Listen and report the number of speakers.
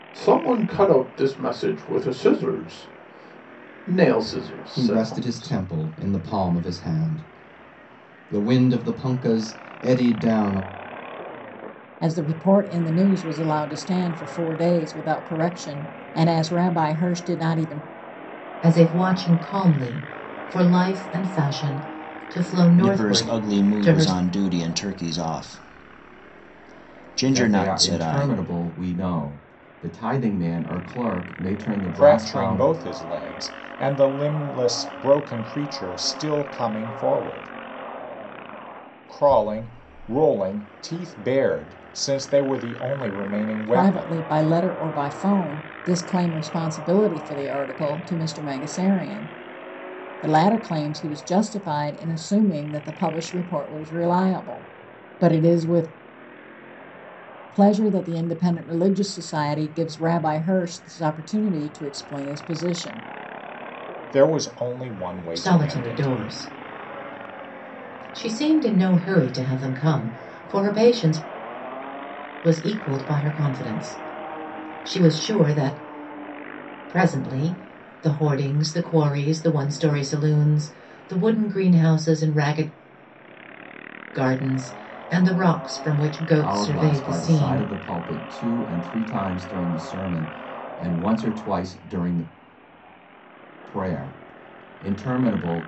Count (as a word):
seven